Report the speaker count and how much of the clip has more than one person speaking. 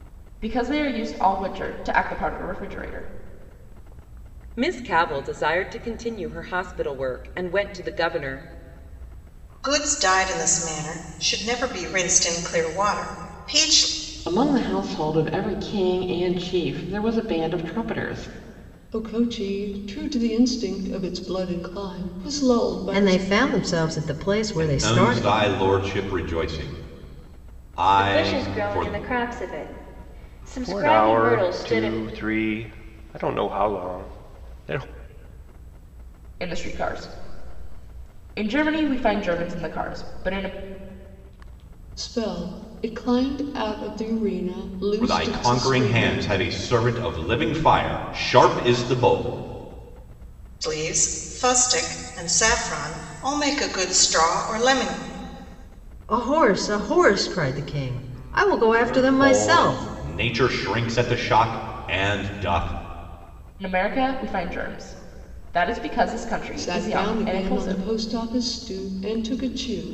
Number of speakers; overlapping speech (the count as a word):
nine, about 11%